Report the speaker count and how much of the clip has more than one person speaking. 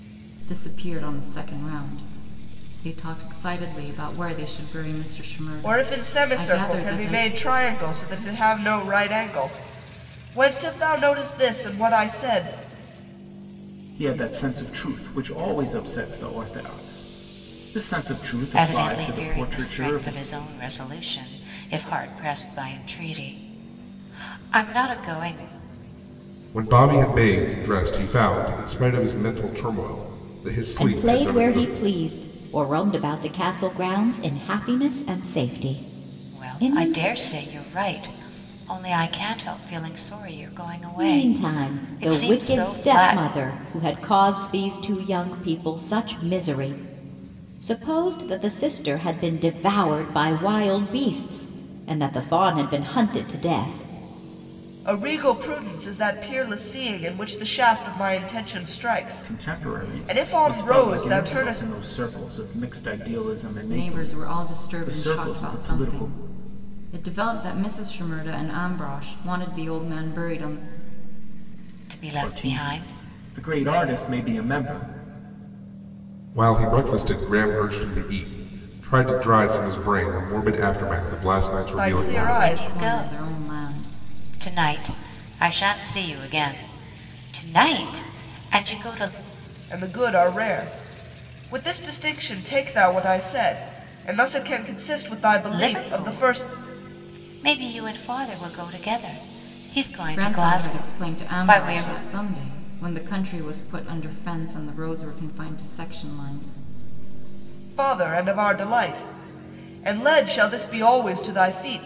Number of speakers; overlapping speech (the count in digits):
6, about 16%